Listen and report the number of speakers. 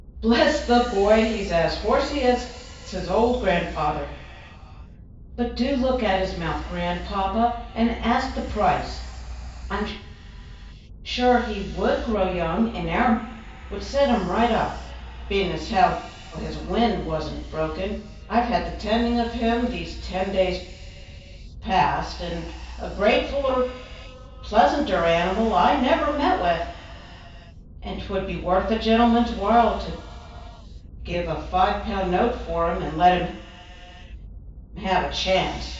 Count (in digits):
1